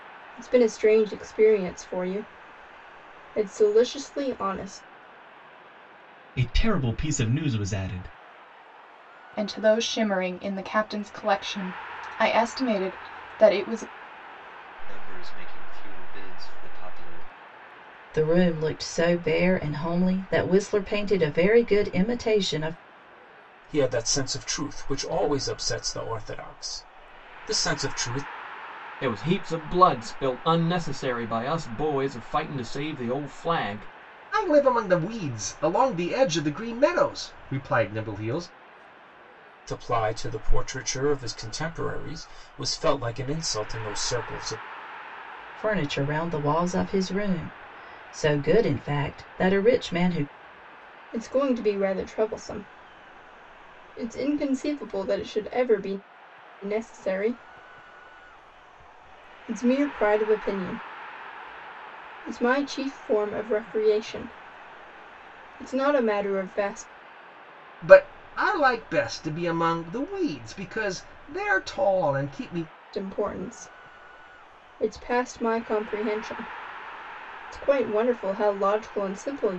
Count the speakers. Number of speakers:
eight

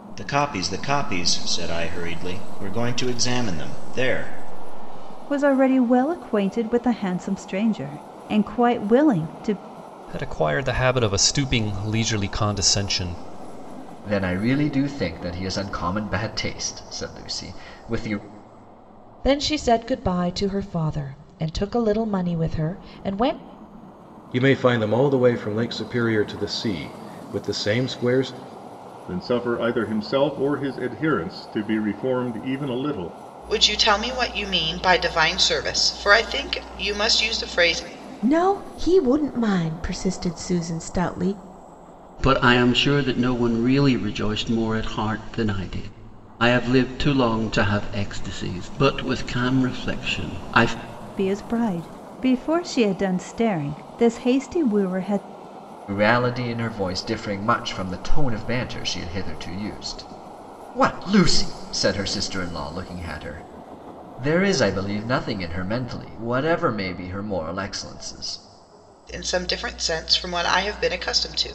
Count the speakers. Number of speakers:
ten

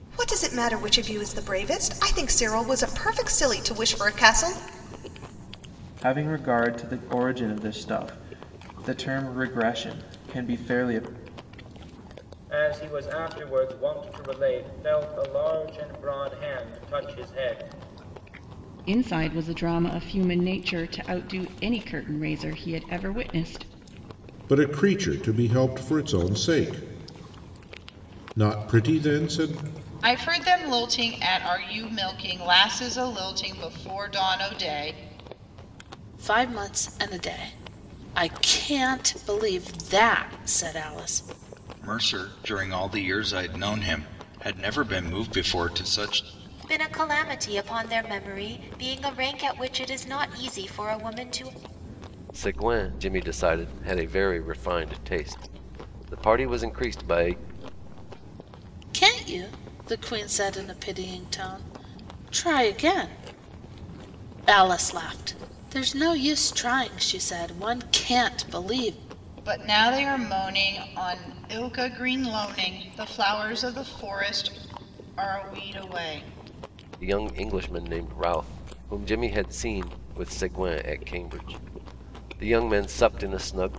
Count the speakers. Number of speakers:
ten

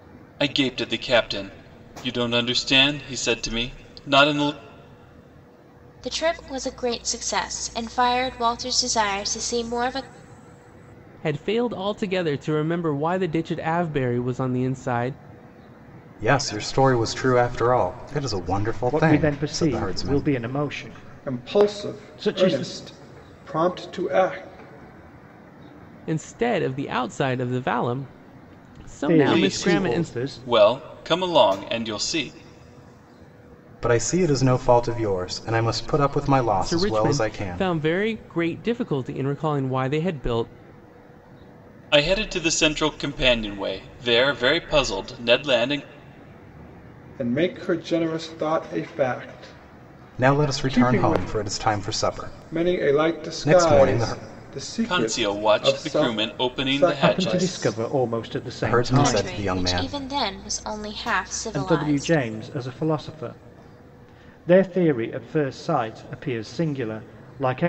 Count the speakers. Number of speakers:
six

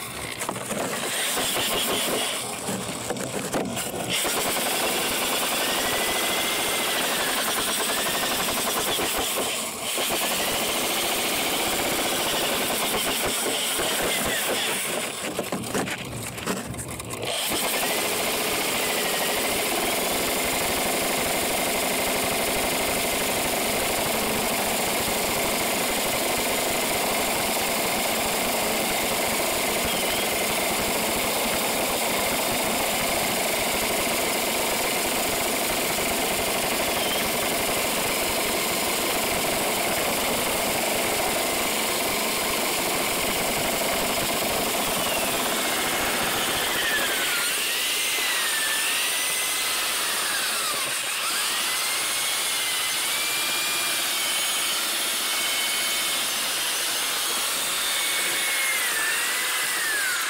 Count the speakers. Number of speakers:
zero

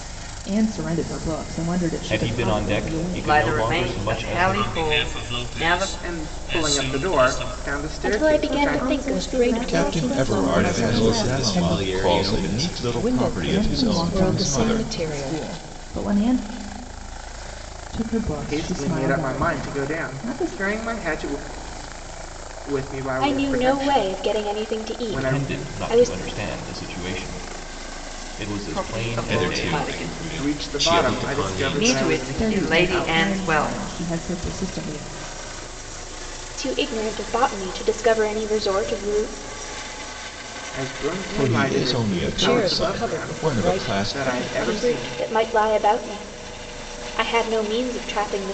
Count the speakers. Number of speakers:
ten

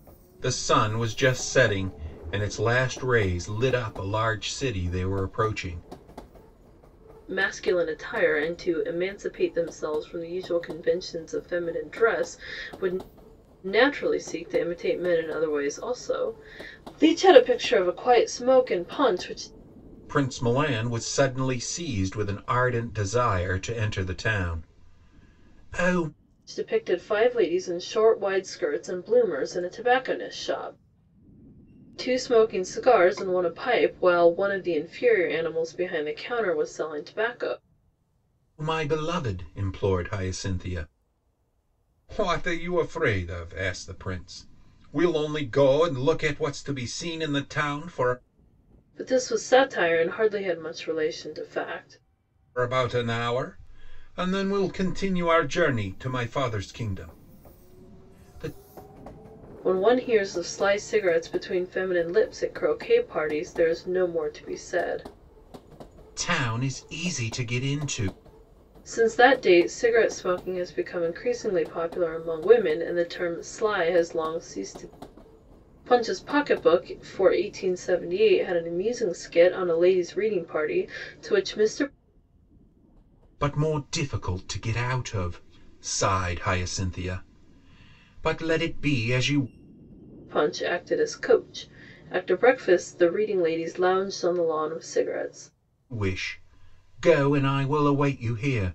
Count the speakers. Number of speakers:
two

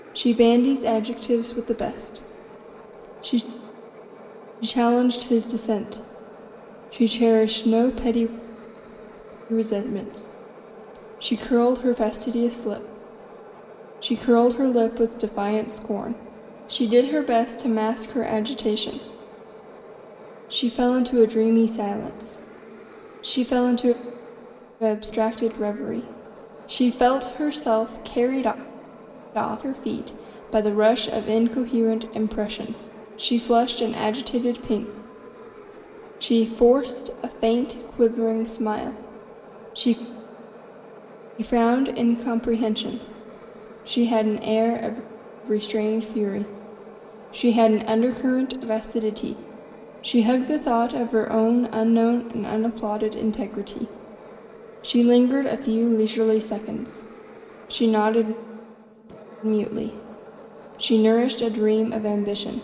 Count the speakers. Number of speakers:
one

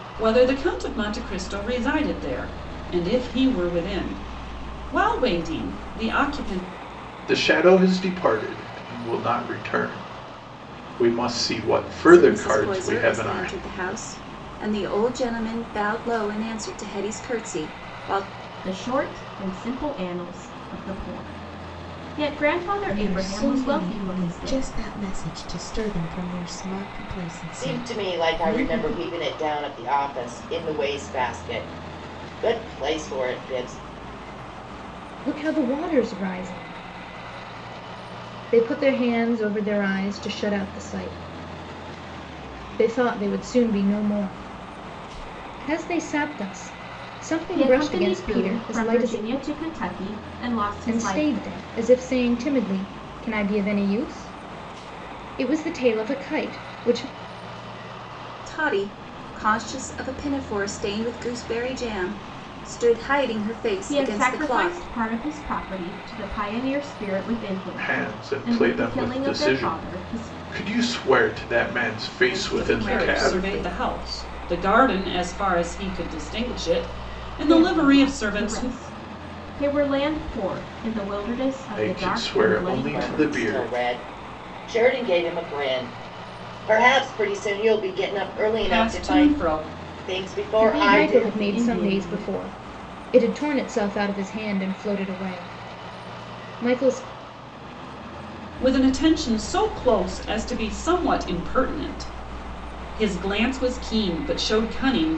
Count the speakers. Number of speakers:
seven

